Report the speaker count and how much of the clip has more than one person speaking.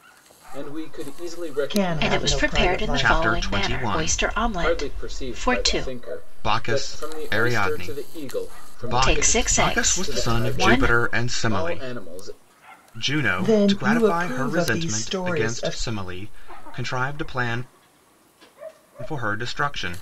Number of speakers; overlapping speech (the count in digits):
4, about 55%